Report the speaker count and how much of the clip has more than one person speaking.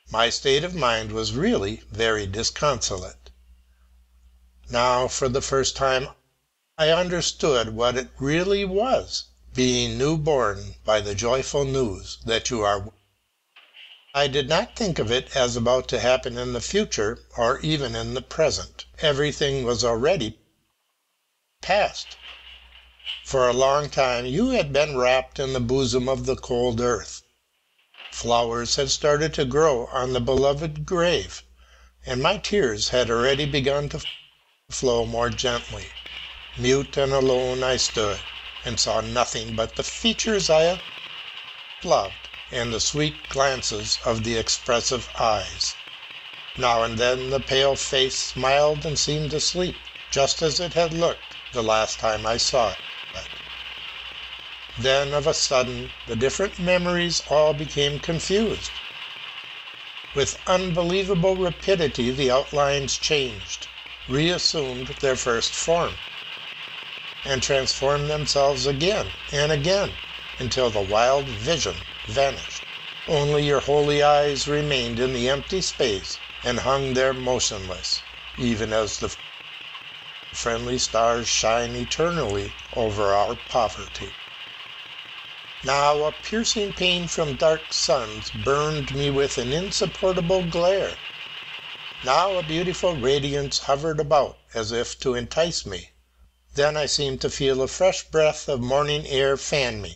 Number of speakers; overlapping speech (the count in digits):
1, no overlap